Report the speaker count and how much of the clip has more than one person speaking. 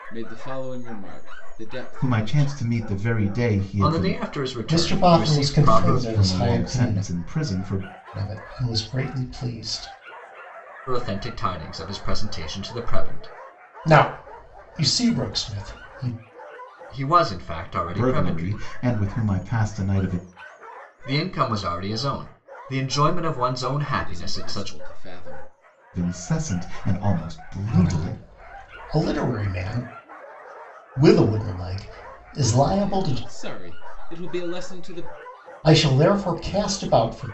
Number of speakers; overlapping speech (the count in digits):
4, about 16%